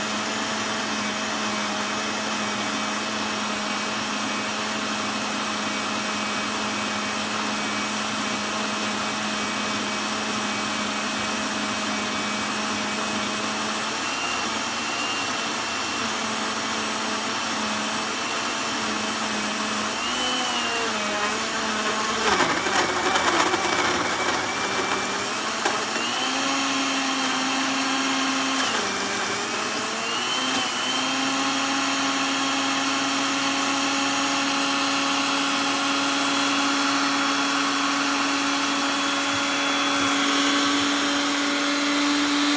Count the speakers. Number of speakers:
0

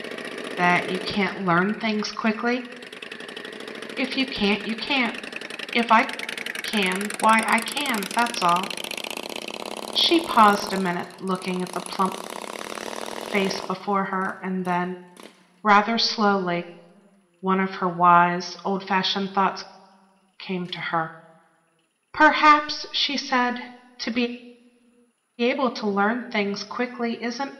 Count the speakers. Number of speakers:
1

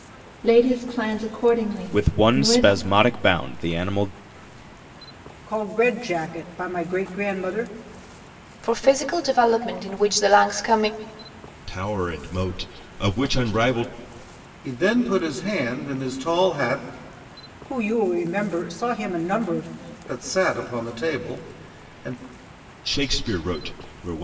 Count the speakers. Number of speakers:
6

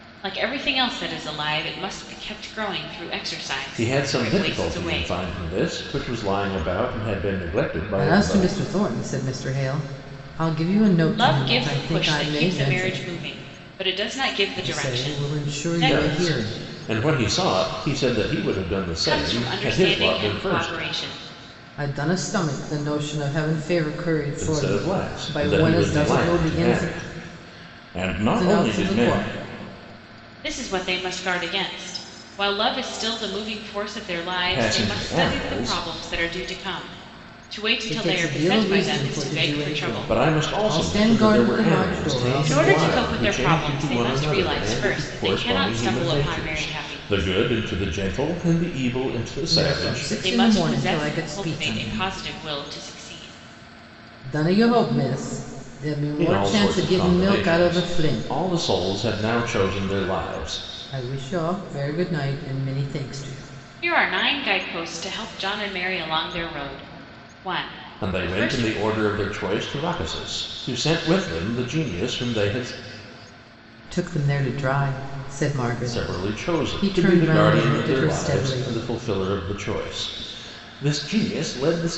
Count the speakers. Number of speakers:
3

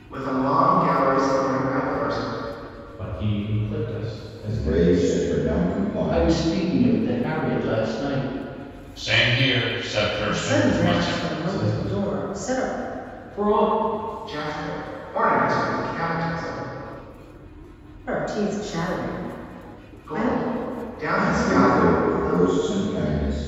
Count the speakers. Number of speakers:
6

